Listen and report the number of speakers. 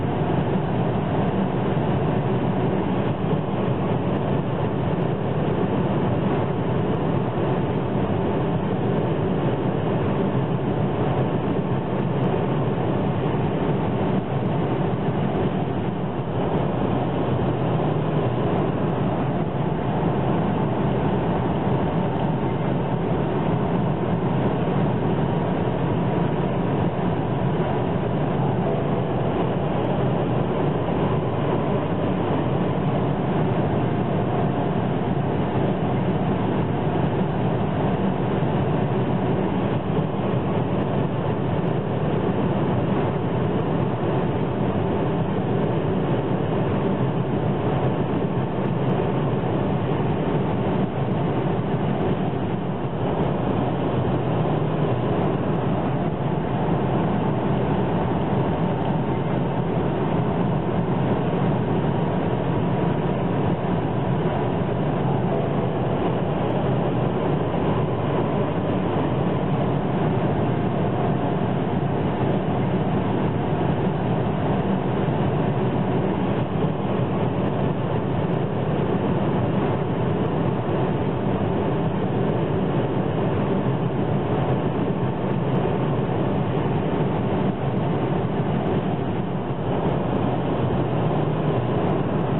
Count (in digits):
0